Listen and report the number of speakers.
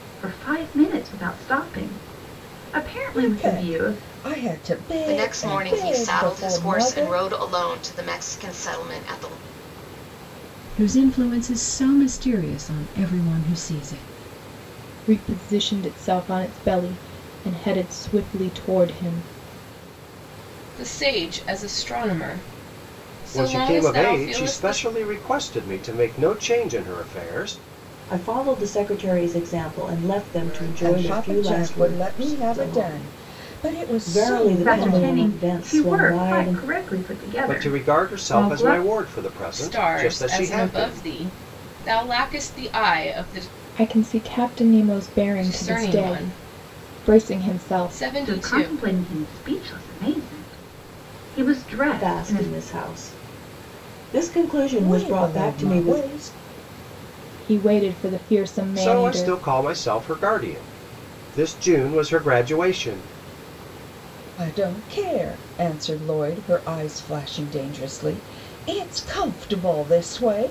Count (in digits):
9